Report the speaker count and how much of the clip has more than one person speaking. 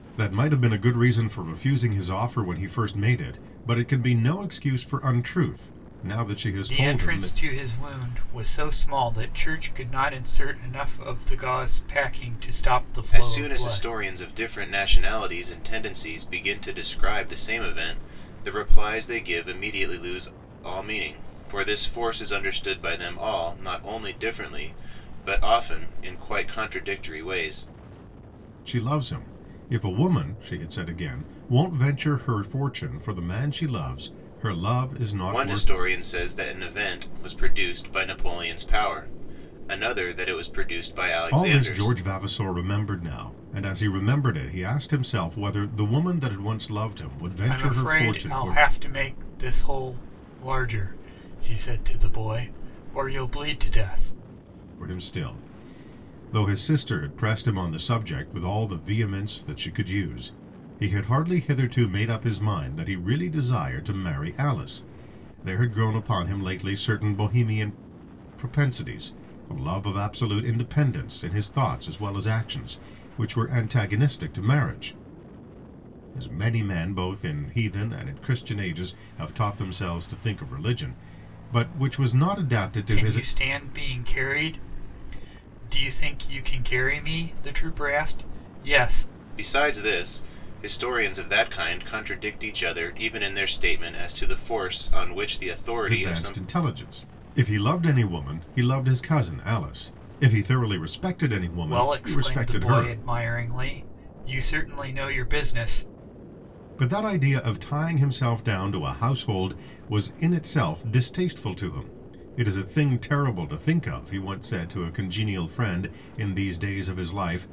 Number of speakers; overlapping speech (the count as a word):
three, about 5%